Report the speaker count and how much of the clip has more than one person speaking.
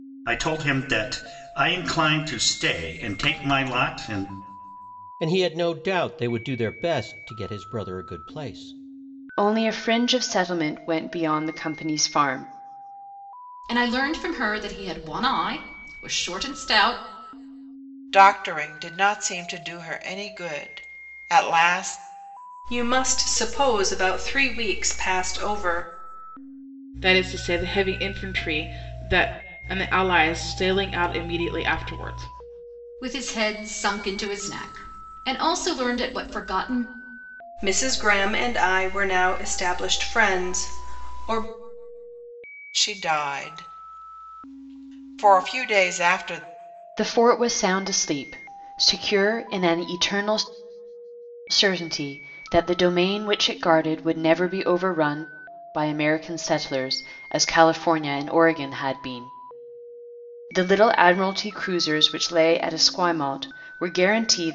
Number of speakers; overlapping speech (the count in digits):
7, no overlap